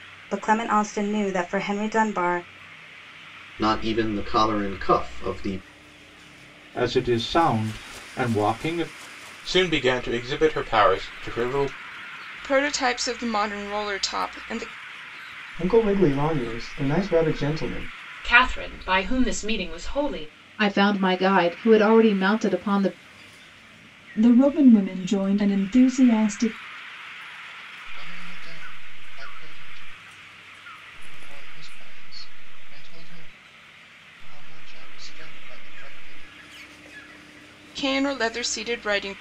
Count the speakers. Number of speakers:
10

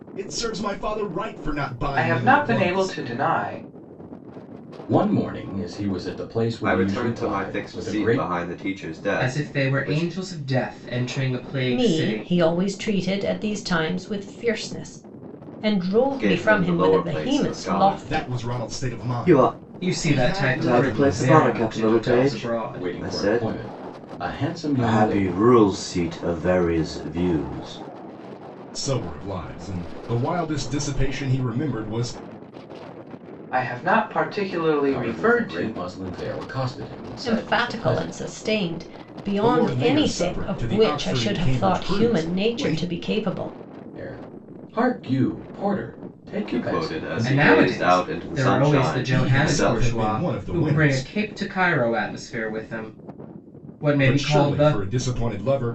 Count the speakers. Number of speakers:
6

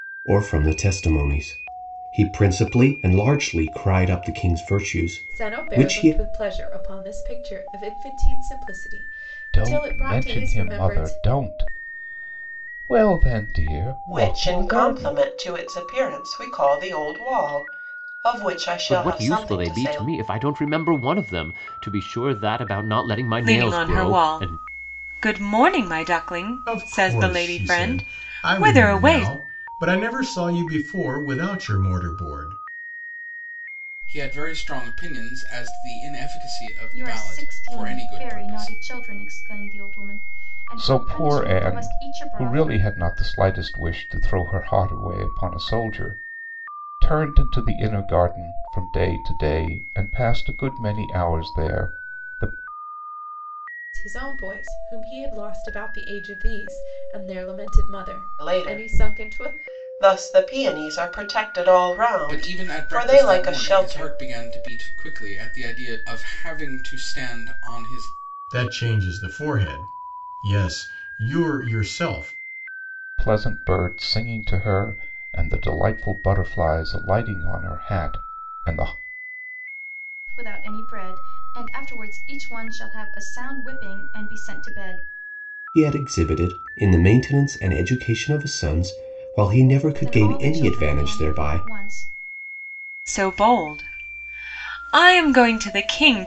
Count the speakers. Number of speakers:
9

